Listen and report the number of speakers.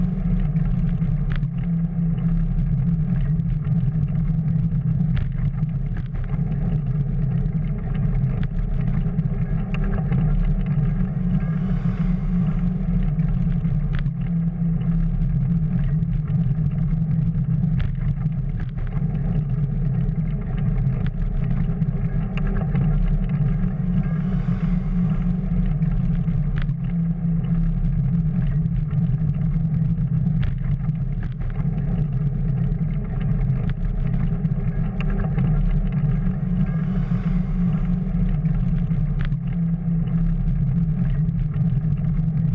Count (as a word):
zero